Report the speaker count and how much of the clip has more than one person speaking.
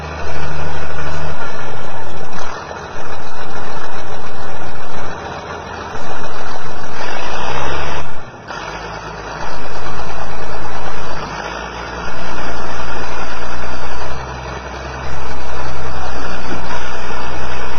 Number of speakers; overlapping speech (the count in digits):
1, no overlap